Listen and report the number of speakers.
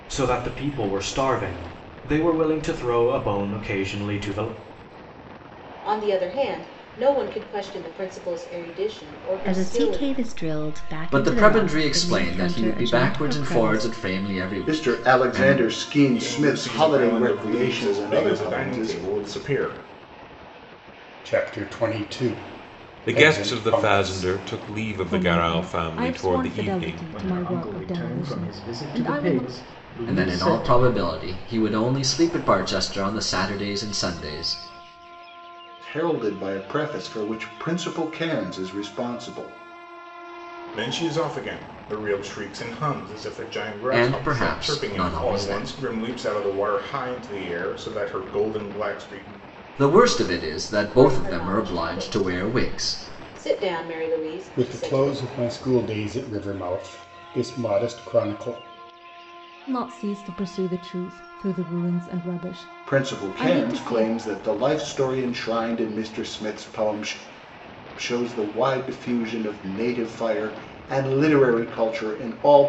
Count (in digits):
10